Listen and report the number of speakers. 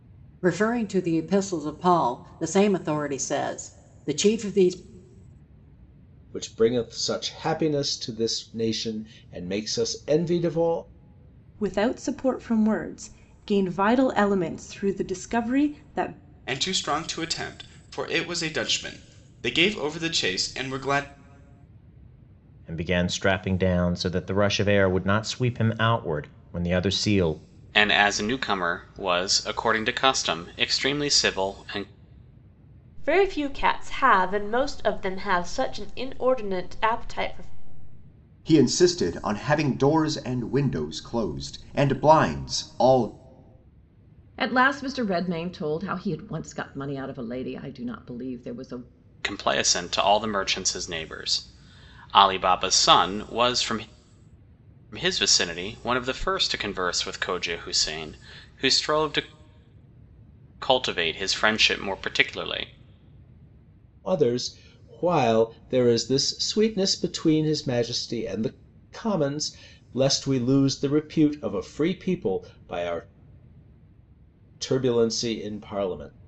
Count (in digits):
9